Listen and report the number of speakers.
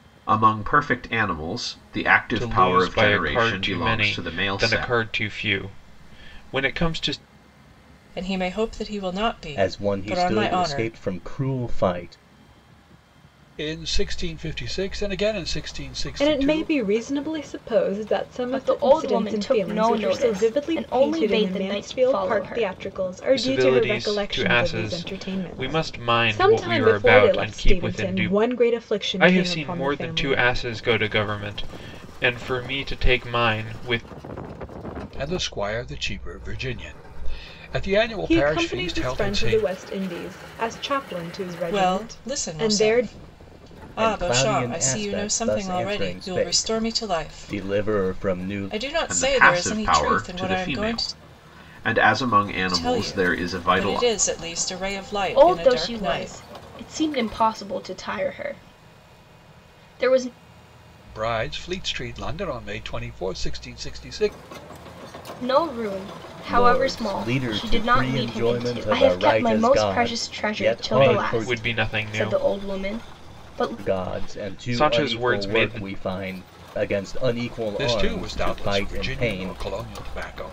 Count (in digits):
7